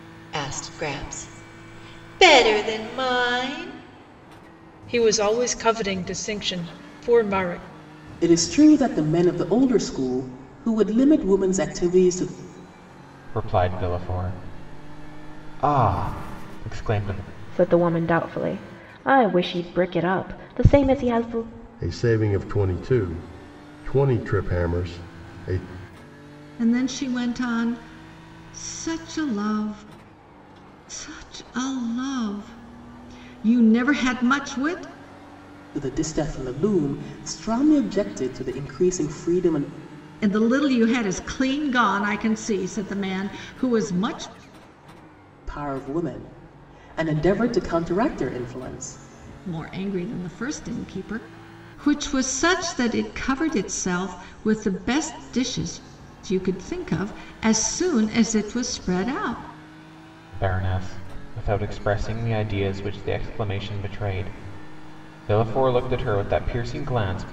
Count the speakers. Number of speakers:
7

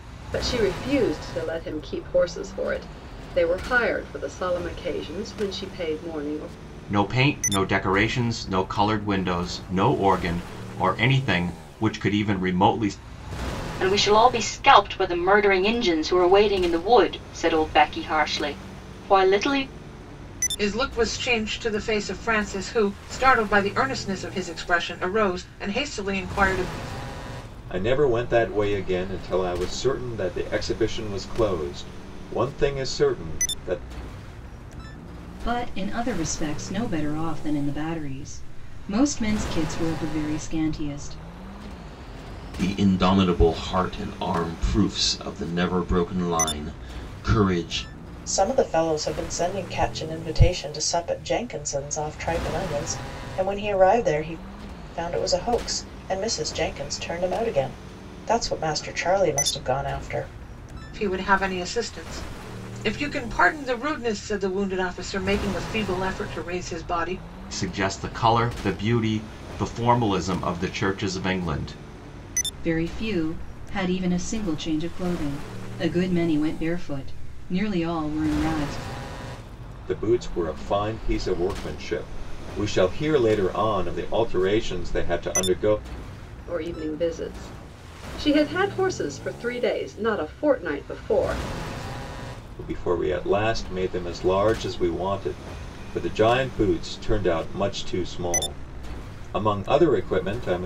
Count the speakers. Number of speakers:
8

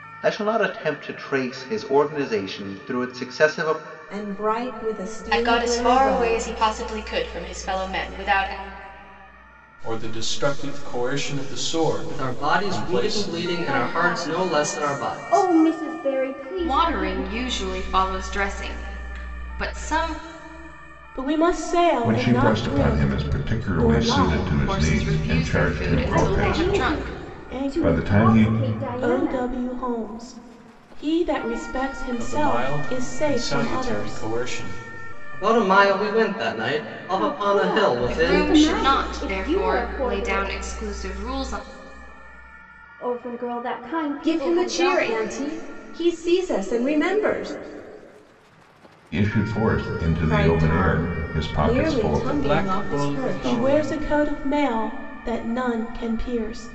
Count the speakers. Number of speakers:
9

